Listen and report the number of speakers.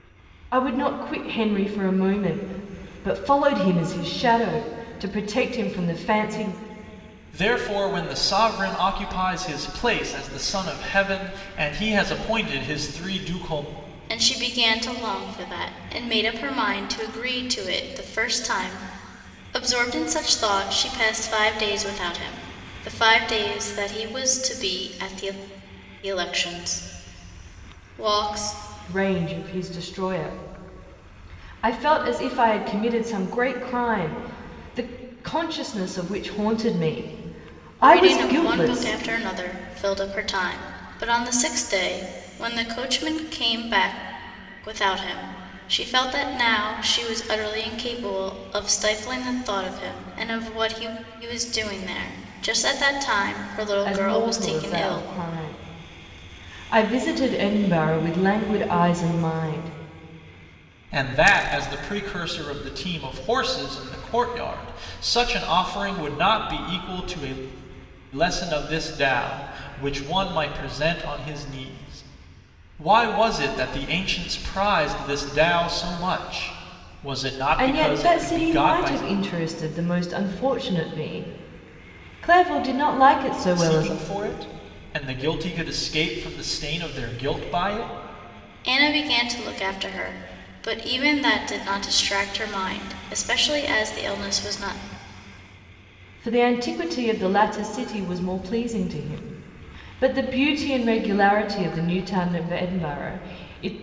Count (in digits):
3